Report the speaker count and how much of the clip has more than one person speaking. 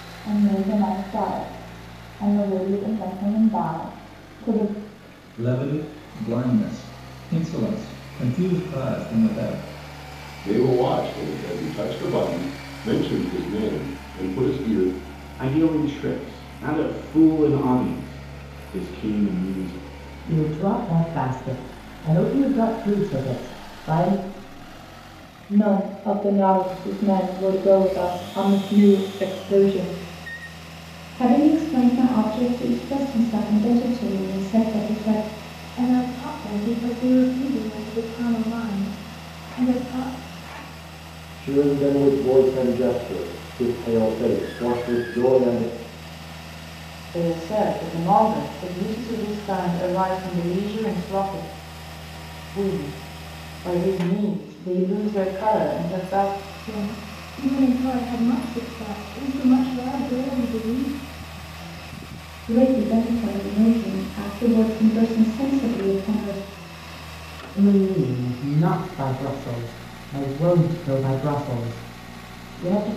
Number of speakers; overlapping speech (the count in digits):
10, no overlap